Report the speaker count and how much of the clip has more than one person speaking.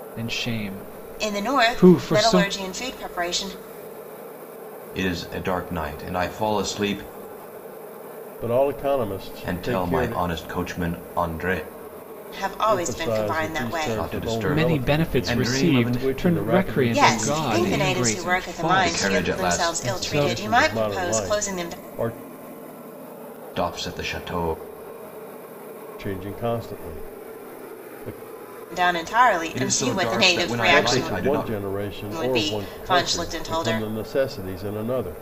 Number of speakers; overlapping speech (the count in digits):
4, about 43%